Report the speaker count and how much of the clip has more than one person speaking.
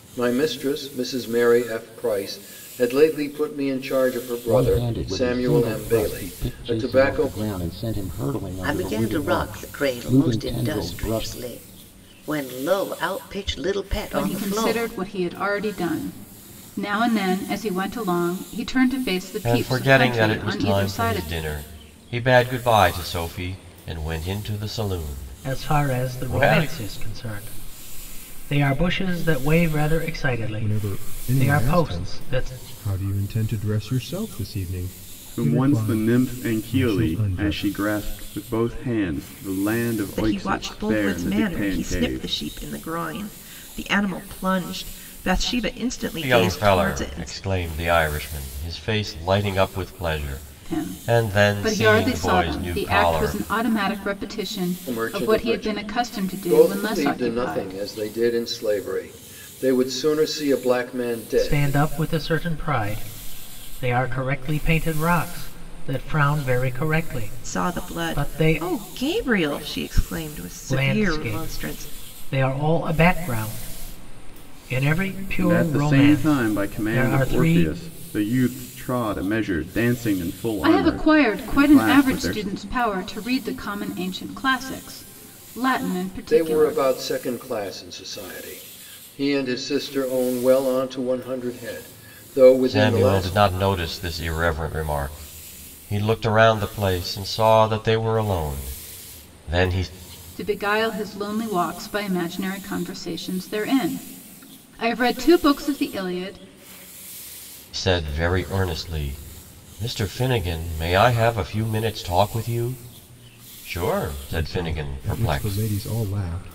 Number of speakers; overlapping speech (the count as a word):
nine, about 29%